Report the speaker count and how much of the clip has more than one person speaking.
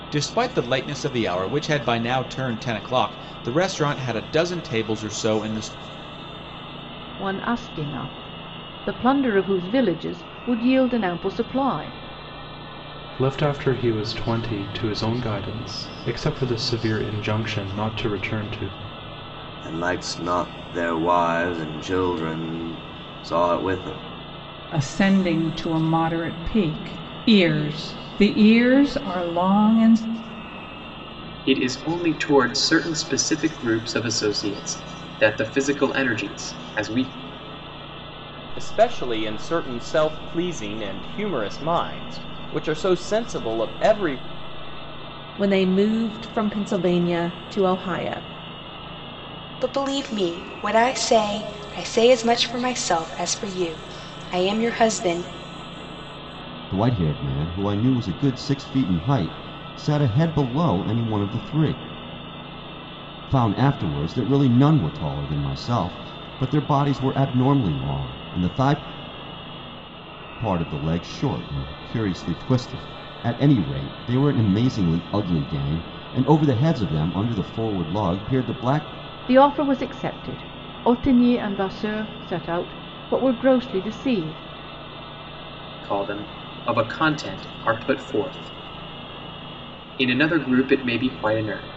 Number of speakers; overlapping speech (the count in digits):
10, no overlap